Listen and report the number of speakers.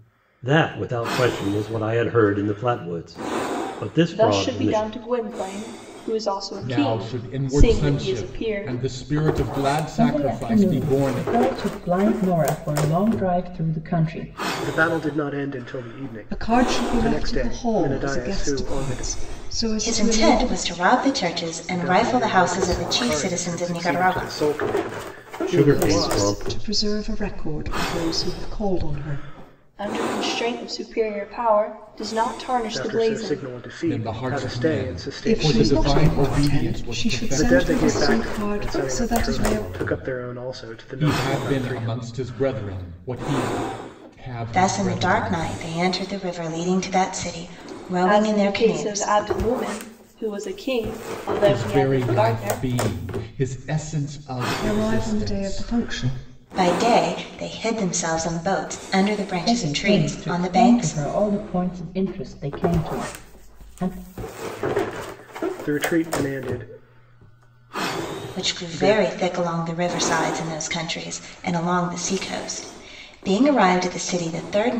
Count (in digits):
7